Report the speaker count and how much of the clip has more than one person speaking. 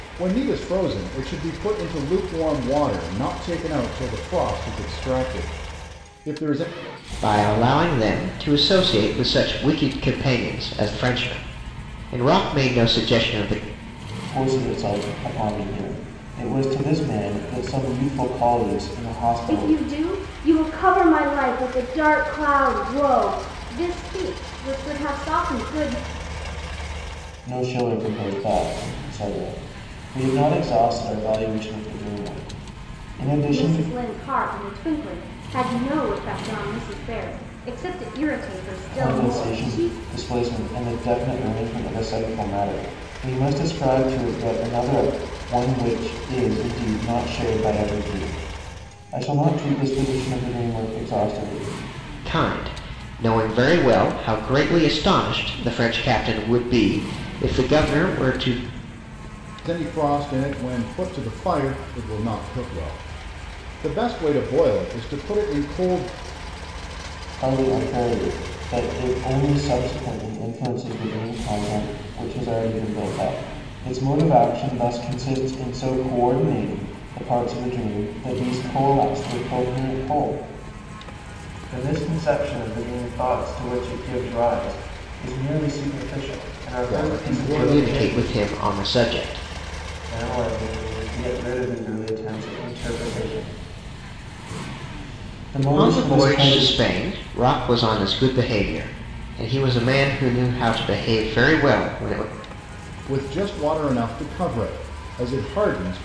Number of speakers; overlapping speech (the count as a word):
four, about 4%